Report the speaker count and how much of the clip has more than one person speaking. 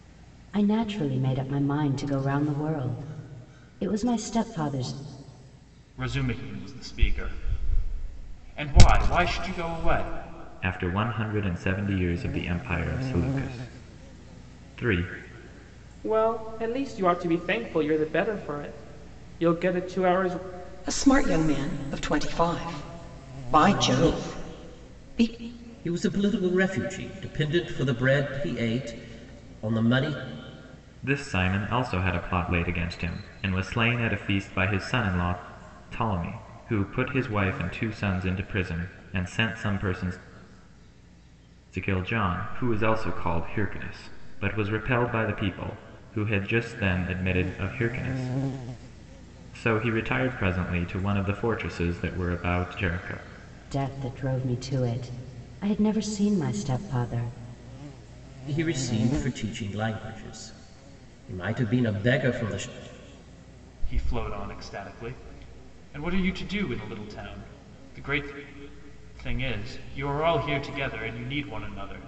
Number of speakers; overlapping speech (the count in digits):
6, no overlap